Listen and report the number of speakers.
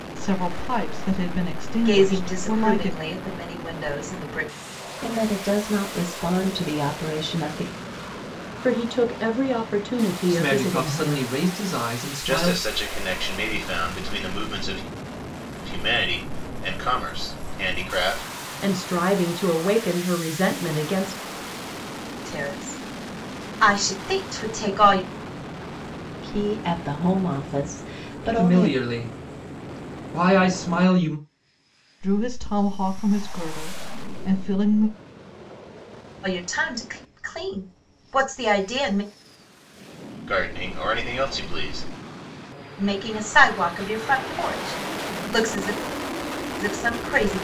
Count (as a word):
six